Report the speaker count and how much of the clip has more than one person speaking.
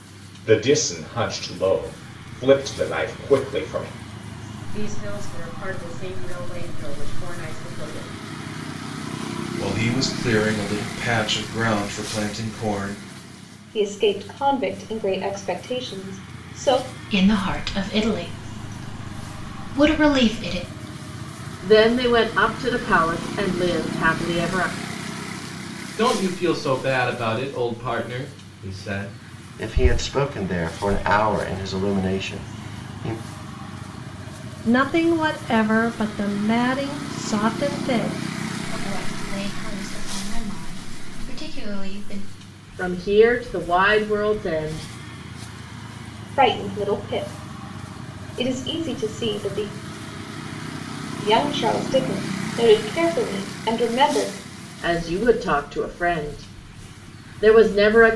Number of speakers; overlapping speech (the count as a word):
ten, no overlap